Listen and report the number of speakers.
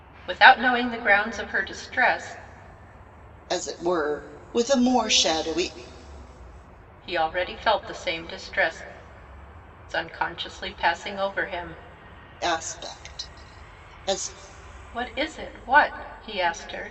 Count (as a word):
two